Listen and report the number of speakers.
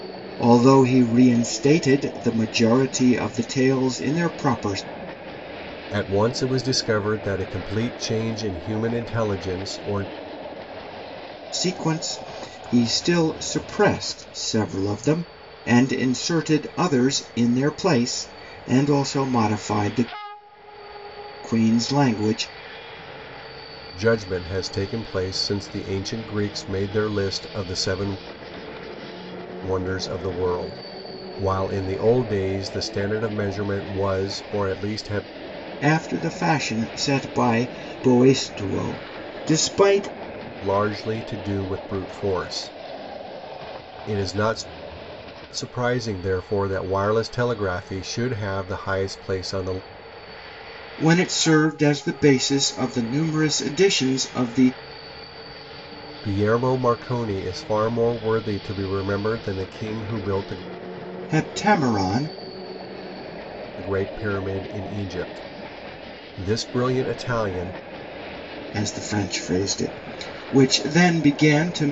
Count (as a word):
two